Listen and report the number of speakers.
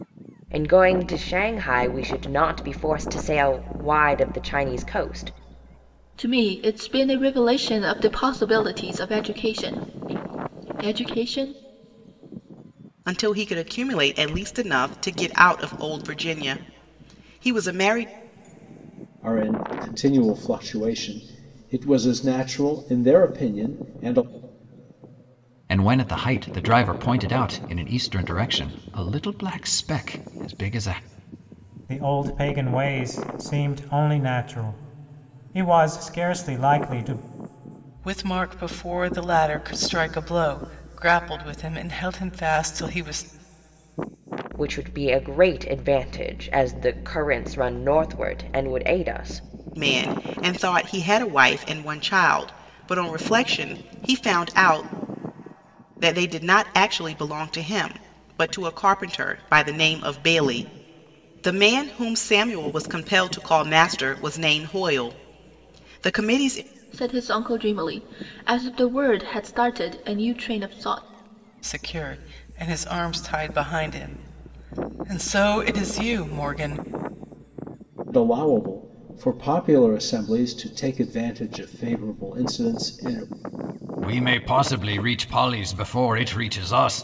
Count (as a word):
seven